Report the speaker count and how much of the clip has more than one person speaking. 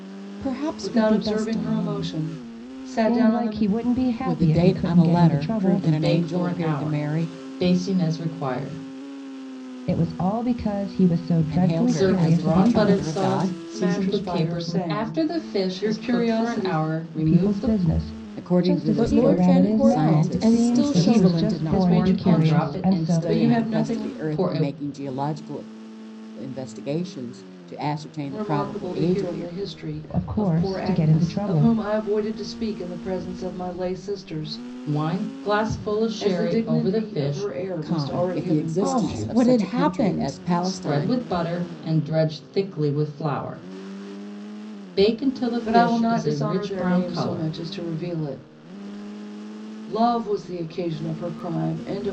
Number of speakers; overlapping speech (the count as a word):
five, about 51%